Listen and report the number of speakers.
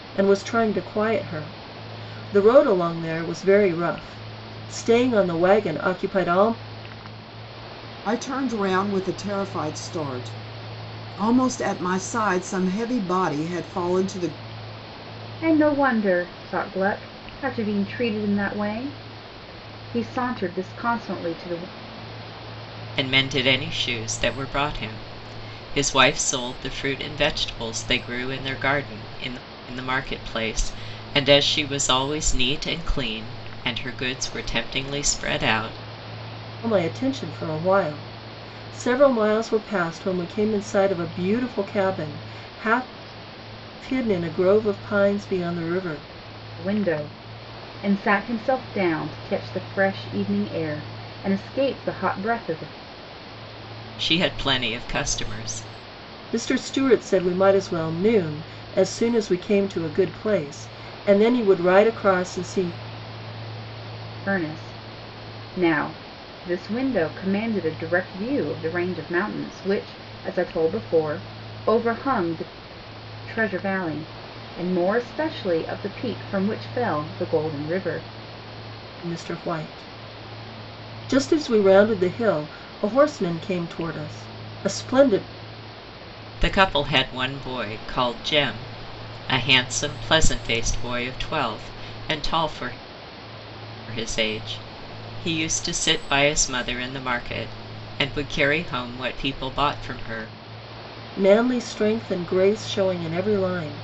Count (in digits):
4